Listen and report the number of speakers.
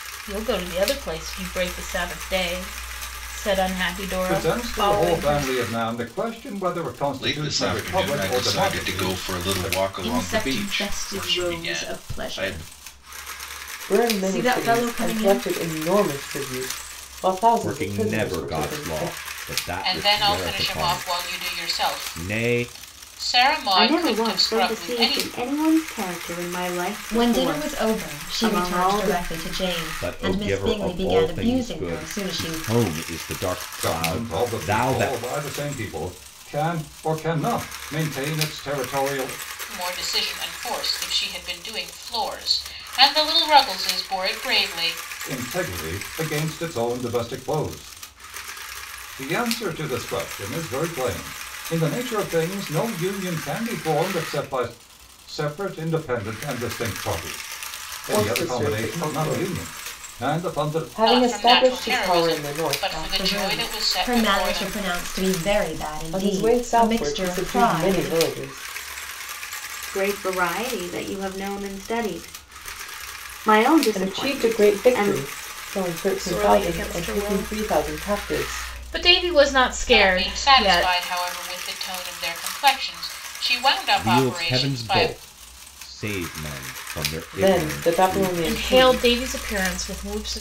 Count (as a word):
nine